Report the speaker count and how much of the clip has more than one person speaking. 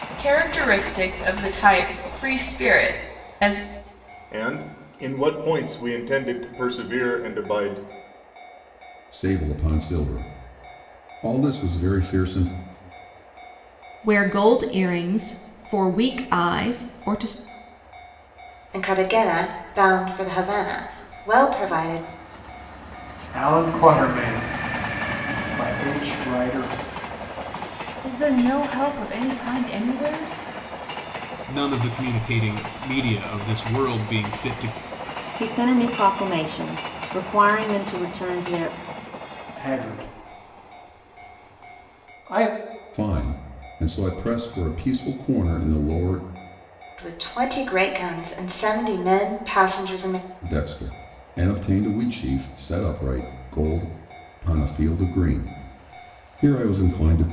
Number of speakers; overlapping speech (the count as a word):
nine, no overlap